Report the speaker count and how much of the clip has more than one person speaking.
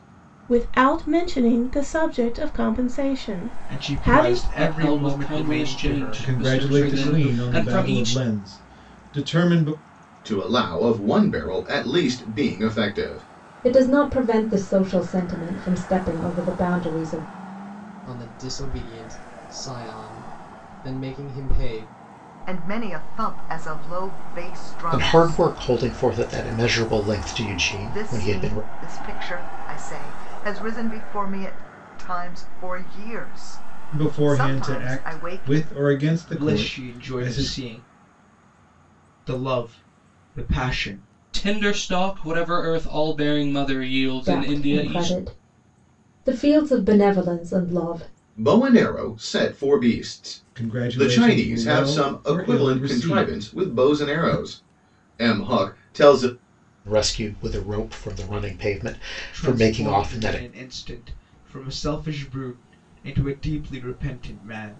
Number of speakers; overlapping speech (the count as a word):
nine, about 23%